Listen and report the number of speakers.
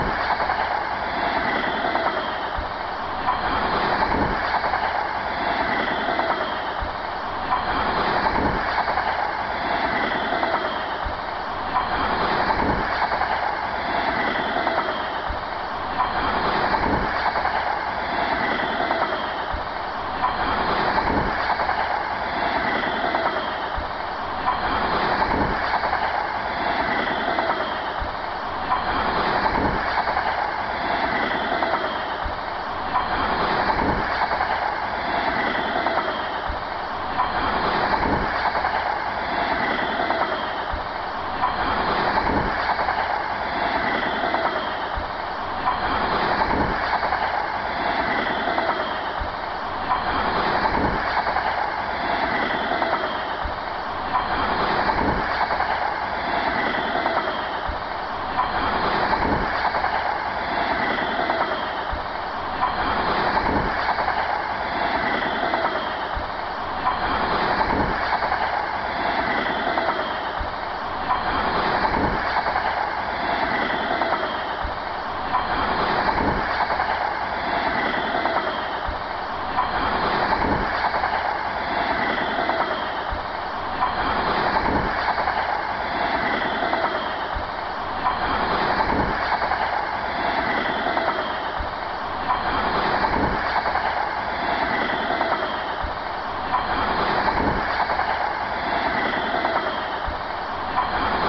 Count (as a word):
zero